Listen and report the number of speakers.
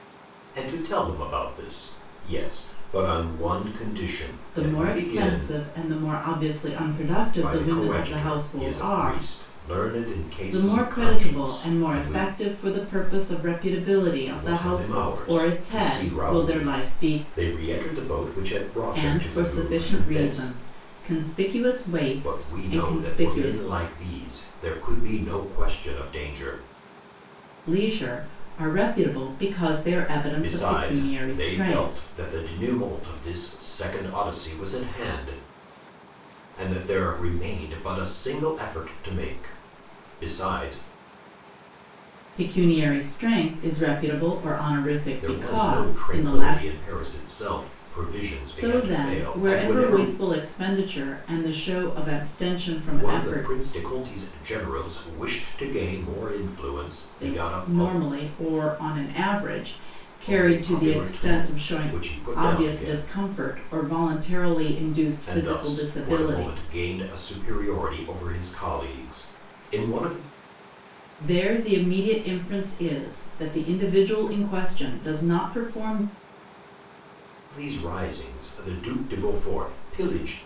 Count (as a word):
two